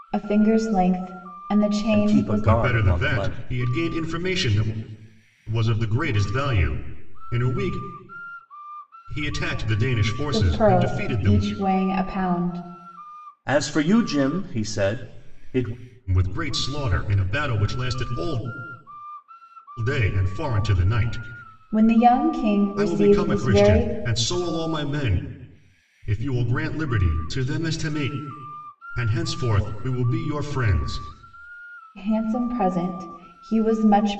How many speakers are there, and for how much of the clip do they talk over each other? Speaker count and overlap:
3, about 11%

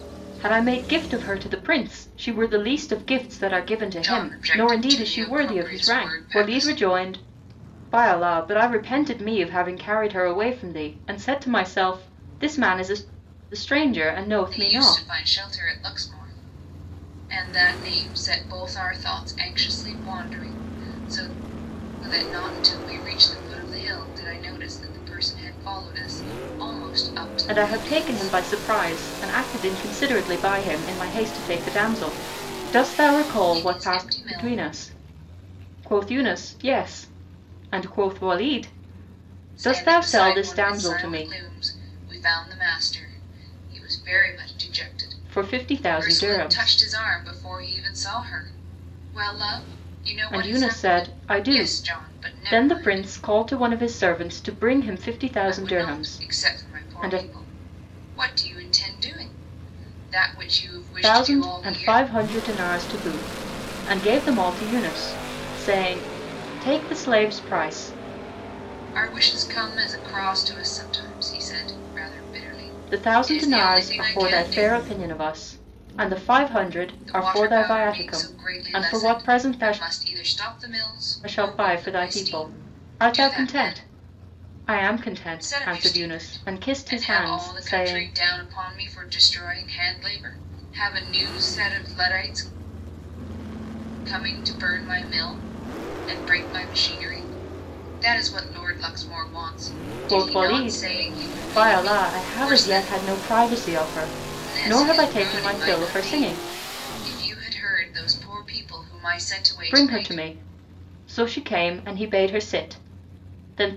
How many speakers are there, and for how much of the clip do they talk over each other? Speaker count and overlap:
2, about 26%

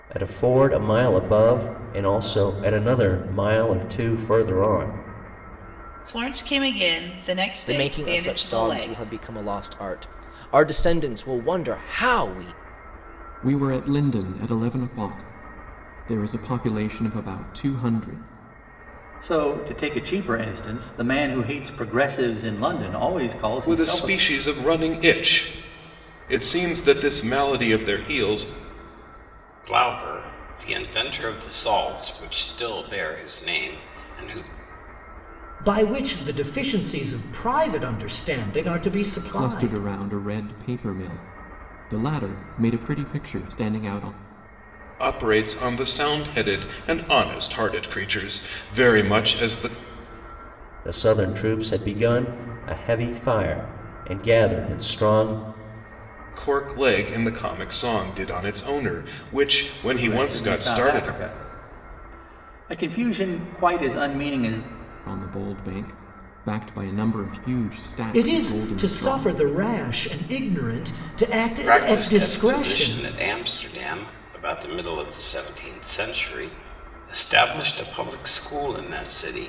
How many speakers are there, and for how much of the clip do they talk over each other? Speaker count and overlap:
8, about 8%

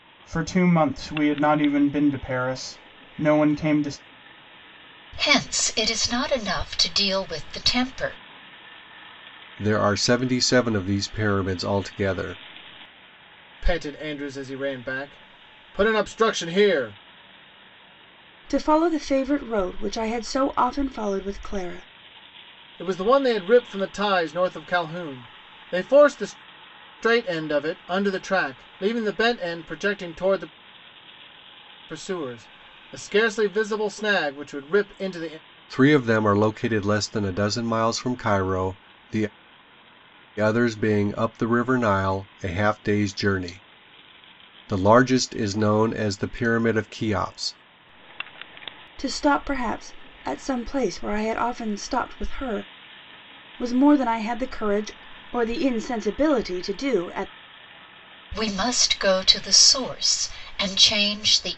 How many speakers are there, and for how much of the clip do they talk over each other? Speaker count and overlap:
5, no overlap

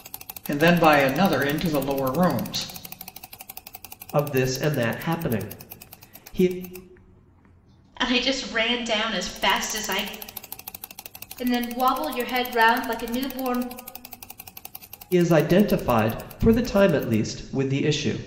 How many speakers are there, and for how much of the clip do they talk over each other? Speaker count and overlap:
4, no overlap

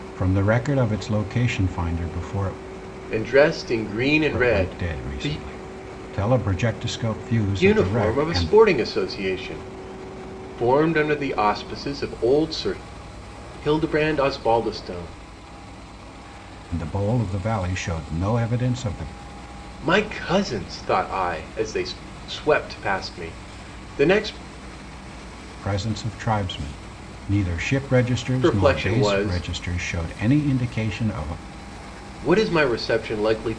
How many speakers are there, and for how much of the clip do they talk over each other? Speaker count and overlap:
2, about 9%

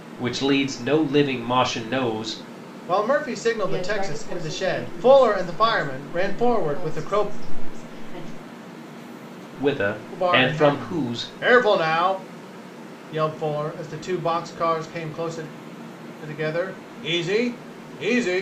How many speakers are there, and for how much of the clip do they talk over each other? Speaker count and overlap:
3, about 26%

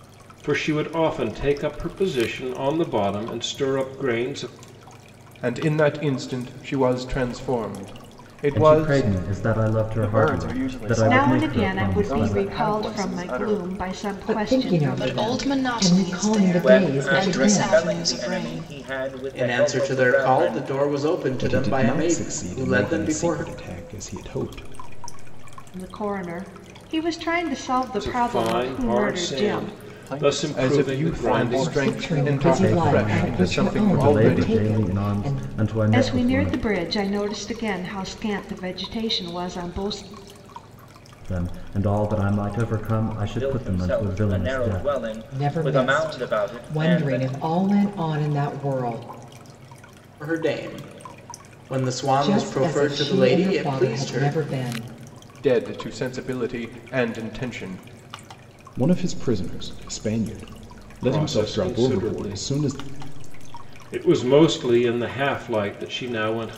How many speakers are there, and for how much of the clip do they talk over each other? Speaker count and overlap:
10, about 42%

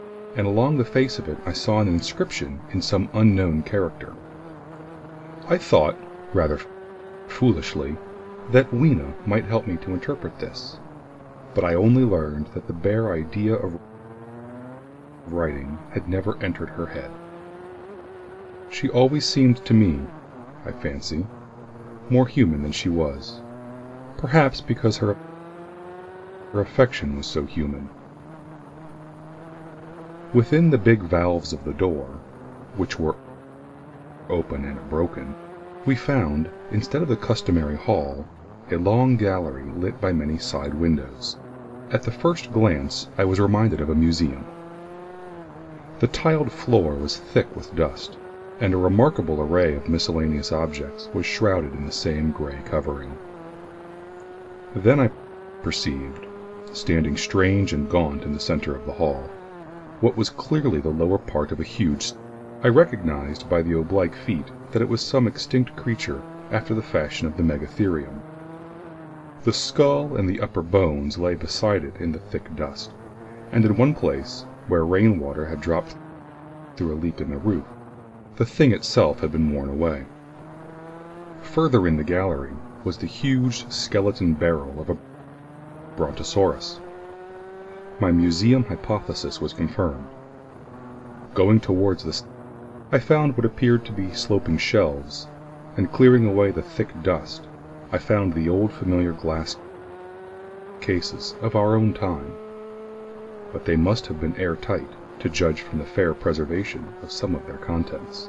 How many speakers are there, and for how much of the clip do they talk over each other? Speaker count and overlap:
1, no overlap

